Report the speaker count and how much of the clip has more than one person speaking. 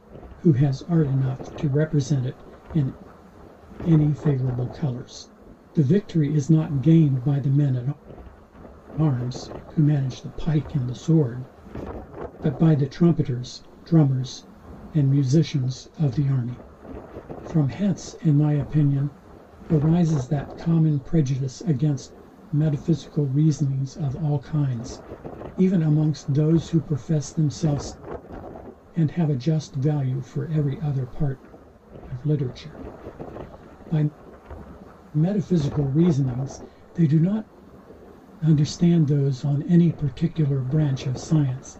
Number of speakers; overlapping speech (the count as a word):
one, no overlap